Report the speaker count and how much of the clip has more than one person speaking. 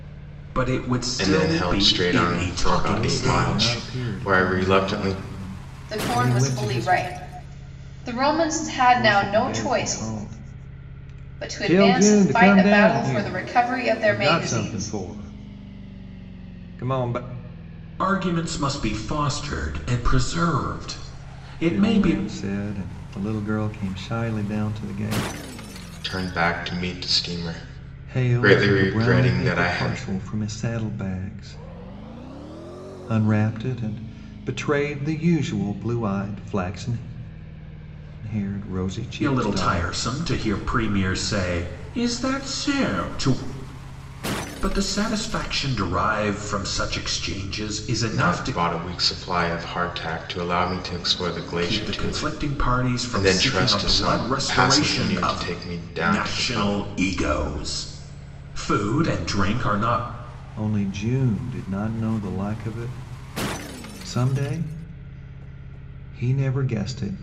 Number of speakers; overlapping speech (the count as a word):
four, about 26%